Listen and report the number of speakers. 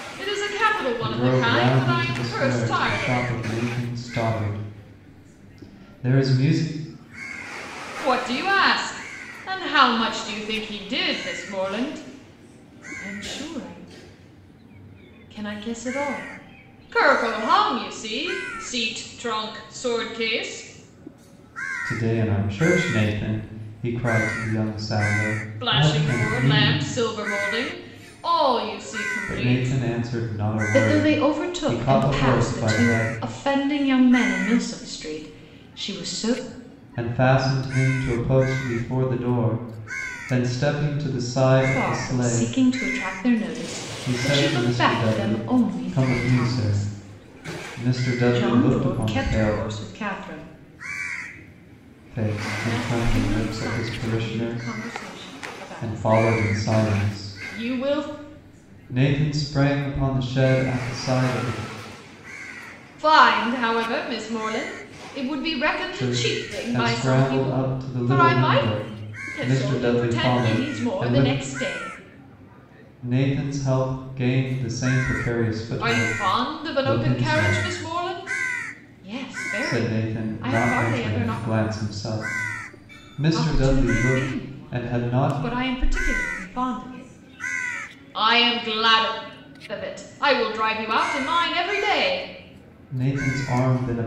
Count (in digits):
2